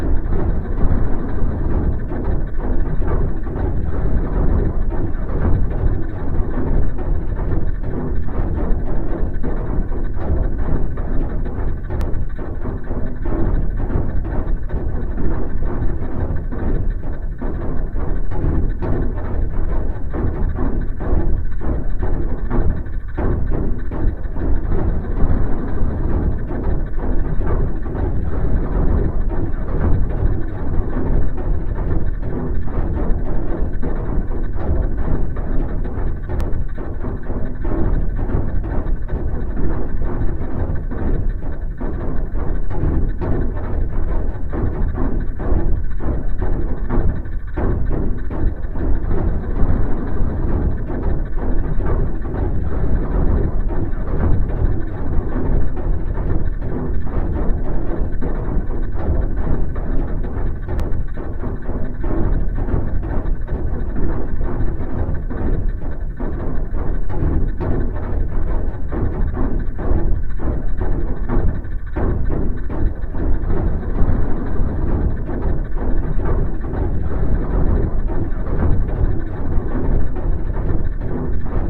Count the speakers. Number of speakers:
zero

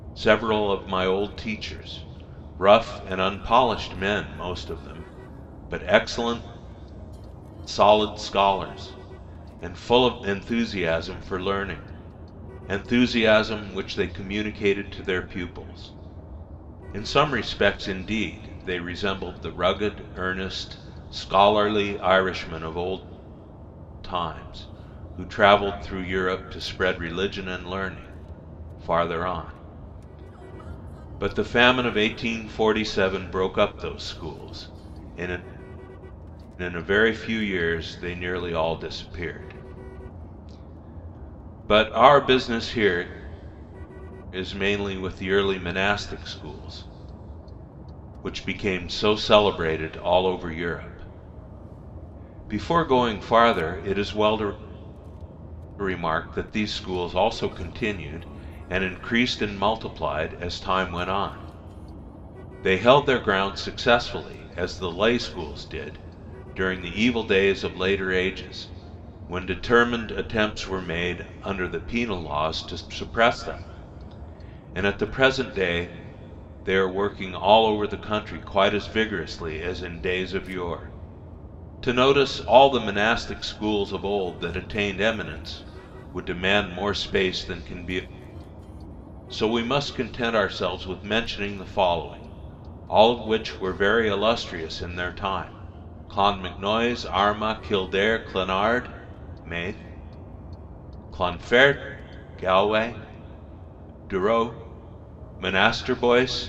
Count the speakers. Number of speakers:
one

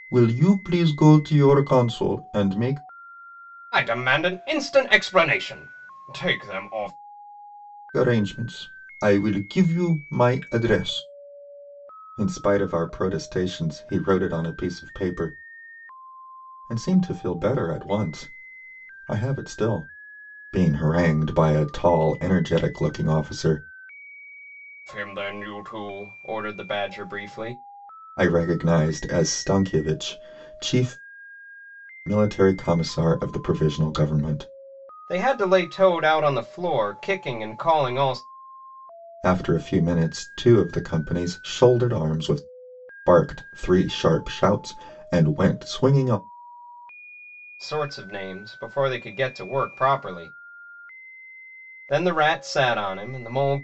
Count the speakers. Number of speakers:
two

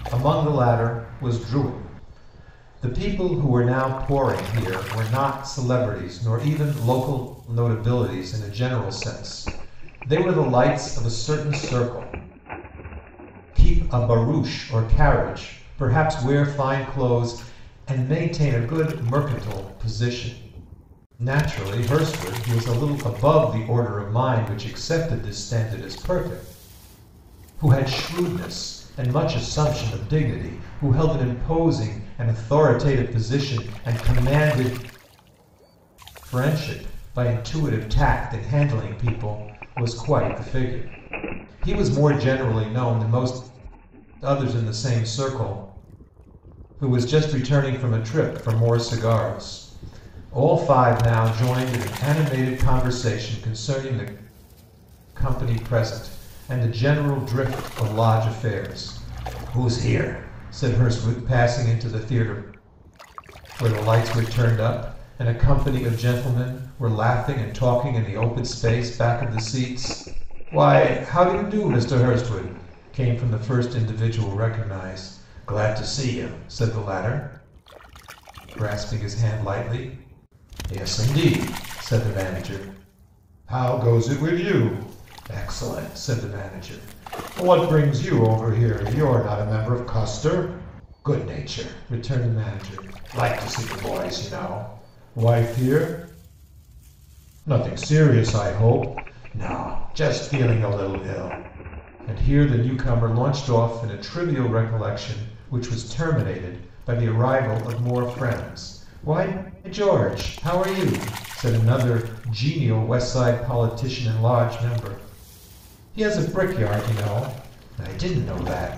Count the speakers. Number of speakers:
one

